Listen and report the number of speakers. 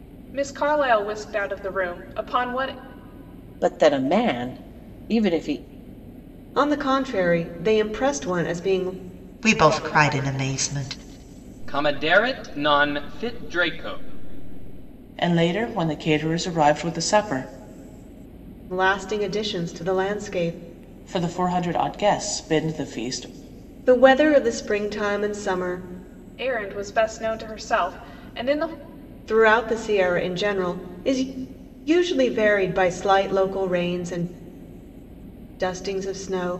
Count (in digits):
6